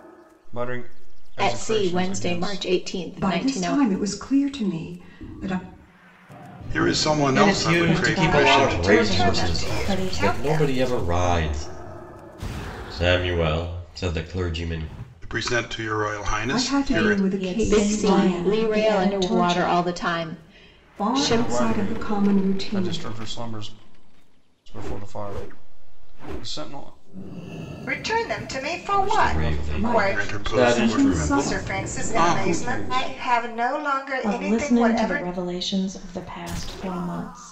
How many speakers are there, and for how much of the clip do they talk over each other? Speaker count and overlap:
7, about 45%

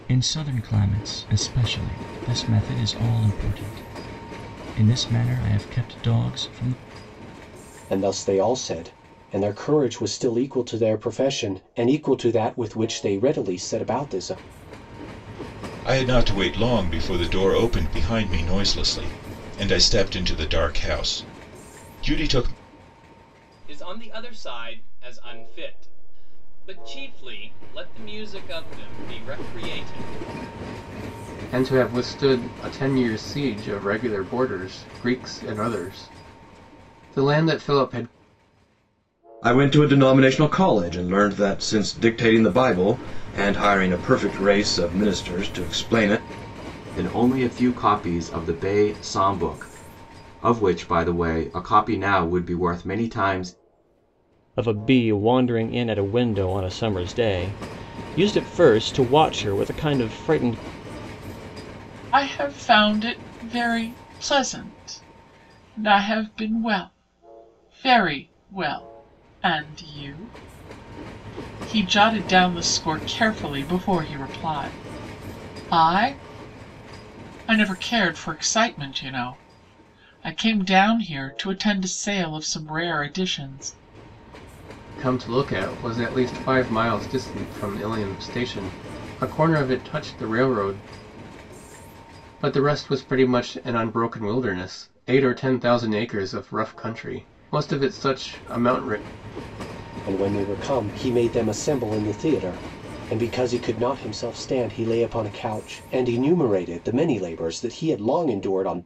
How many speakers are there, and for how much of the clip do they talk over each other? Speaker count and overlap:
9, no overlap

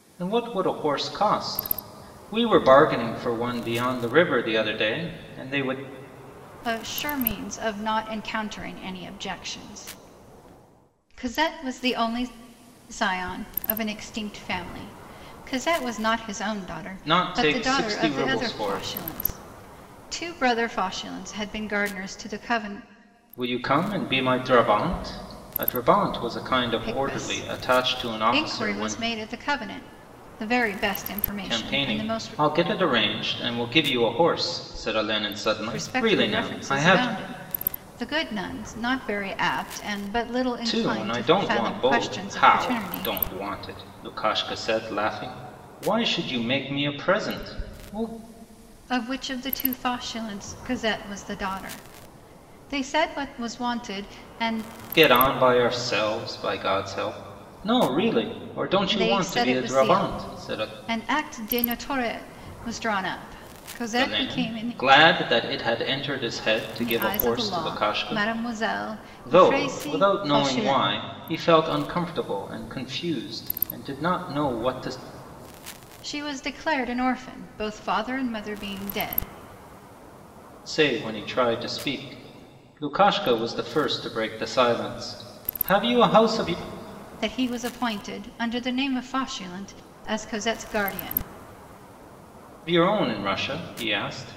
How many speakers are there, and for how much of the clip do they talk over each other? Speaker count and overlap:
2, about 16%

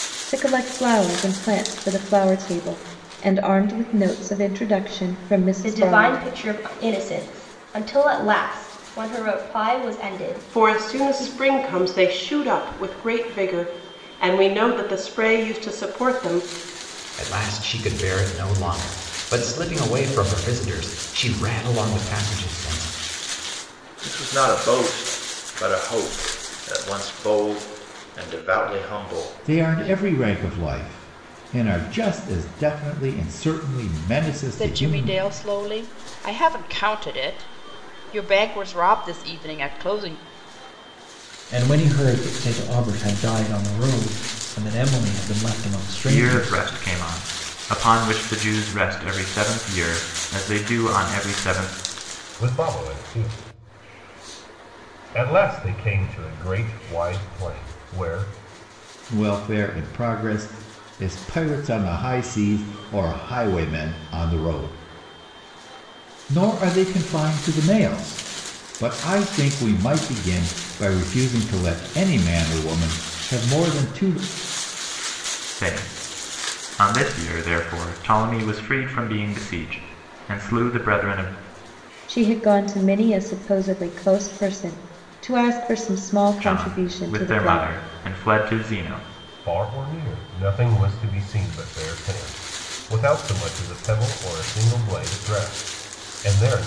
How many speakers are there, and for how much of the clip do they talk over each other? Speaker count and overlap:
10, about 5%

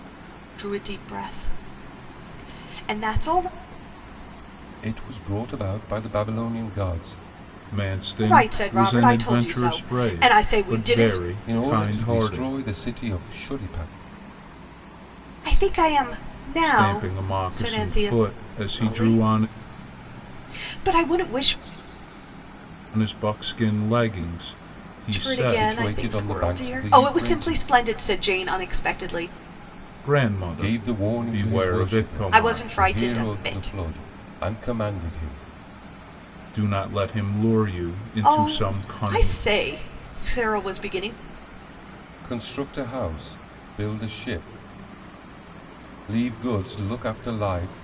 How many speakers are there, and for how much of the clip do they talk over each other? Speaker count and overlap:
3, about 28%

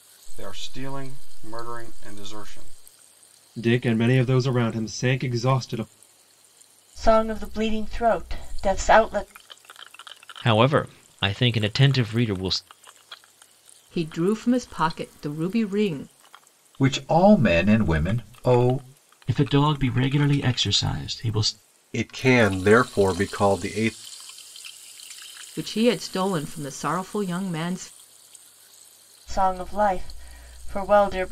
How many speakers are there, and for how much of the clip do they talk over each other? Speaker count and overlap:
8, no overlap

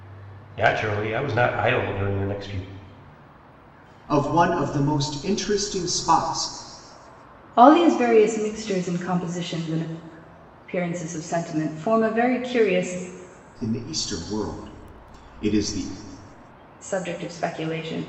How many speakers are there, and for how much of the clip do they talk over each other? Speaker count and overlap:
3, no overlap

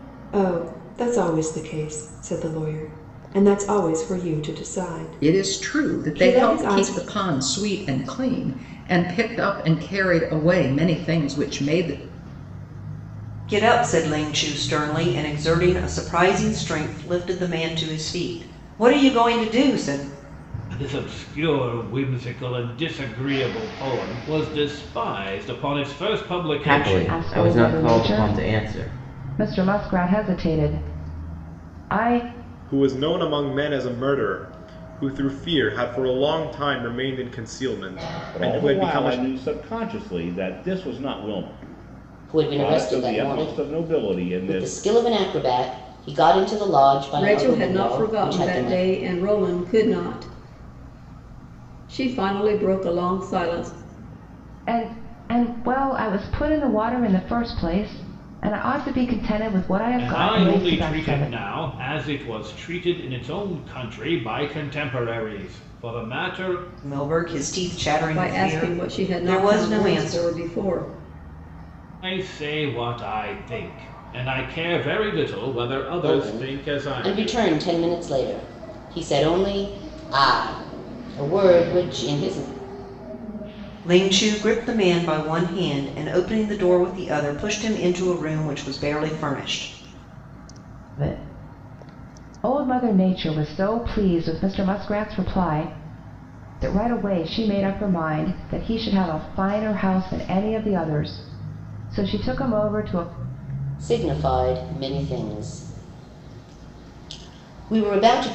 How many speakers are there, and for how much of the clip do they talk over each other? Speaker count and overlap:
10, about 13%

